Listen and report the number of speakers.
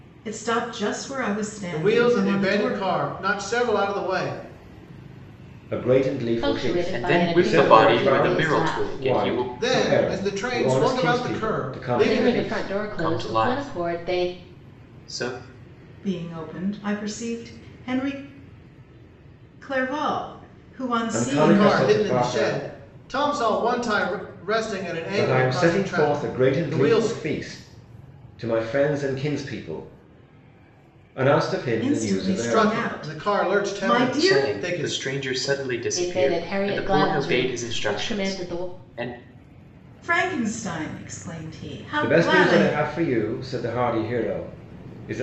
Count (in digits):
5